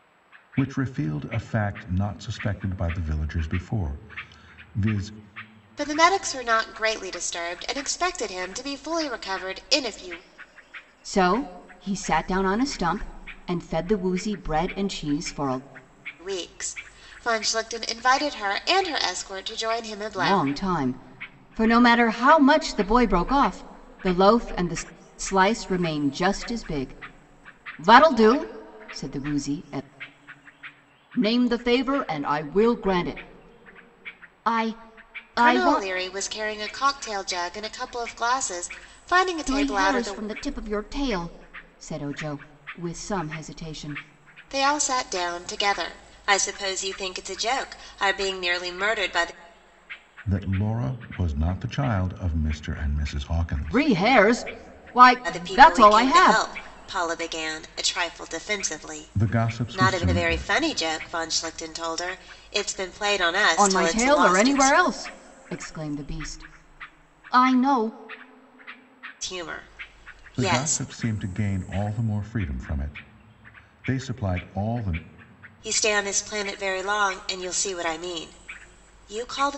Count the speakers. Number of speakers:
3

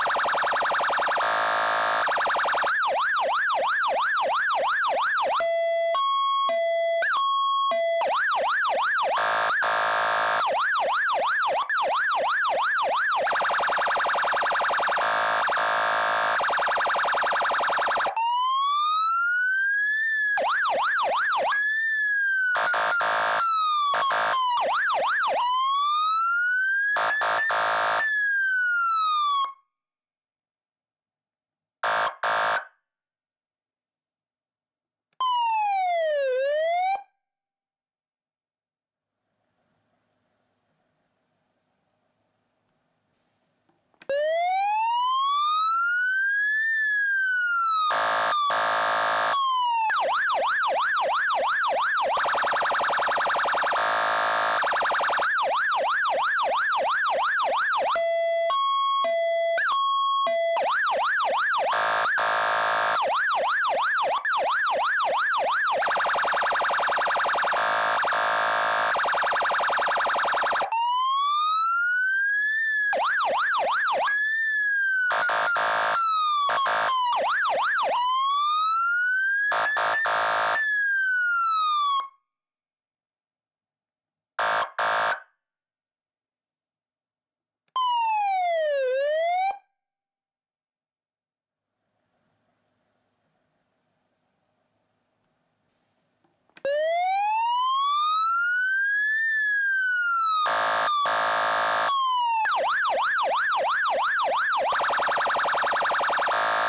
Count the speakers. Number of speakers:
0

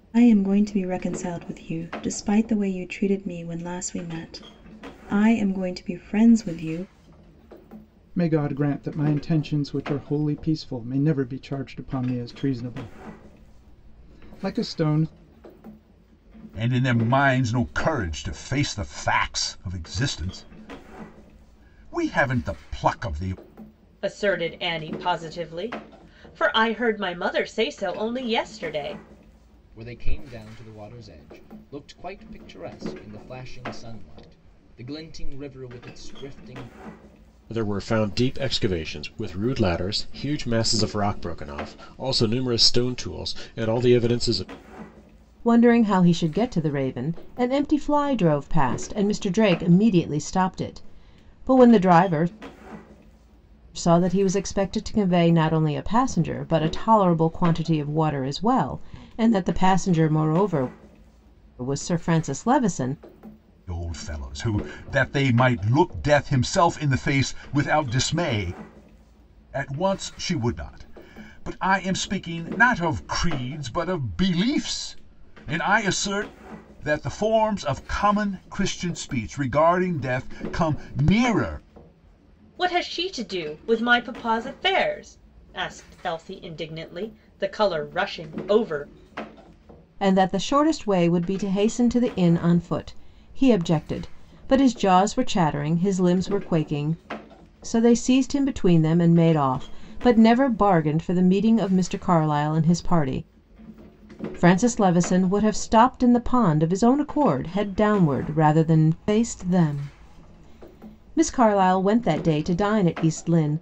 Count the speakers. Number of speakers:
7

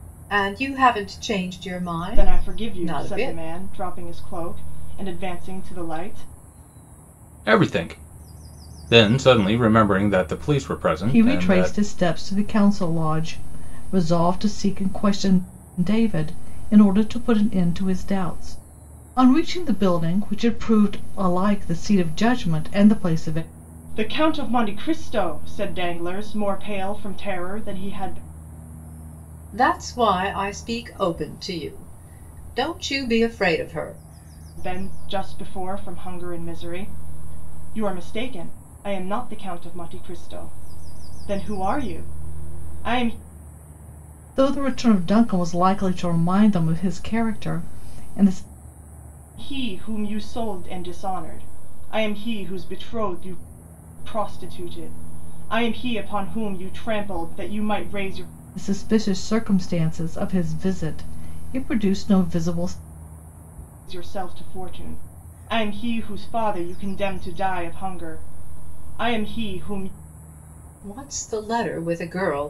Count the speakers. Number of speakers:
4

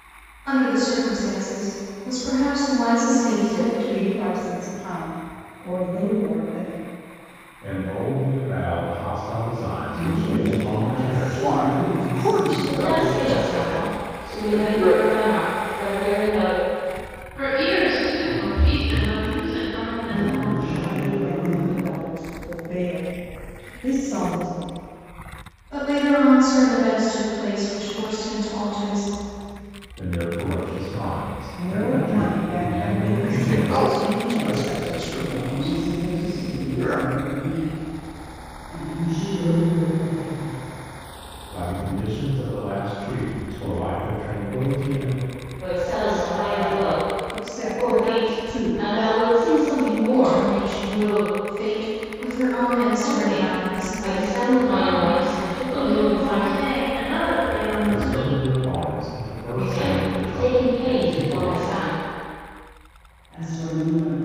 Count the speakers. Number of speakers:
7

